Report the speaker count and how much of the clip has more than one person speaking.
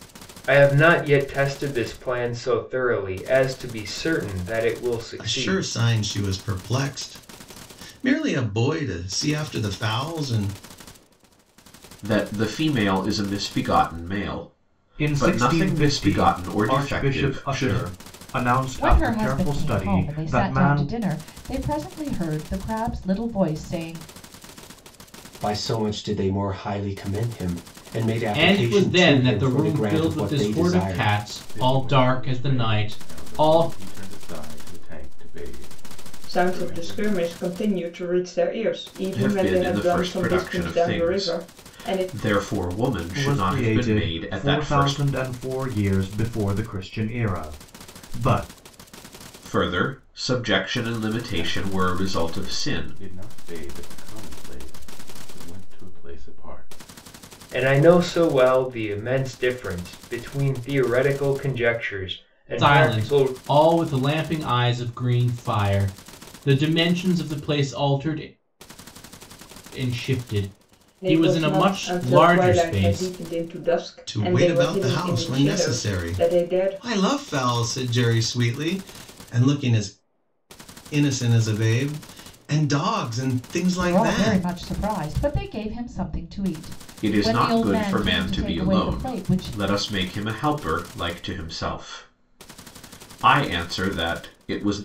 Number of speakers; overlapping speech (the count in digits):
9, about 29%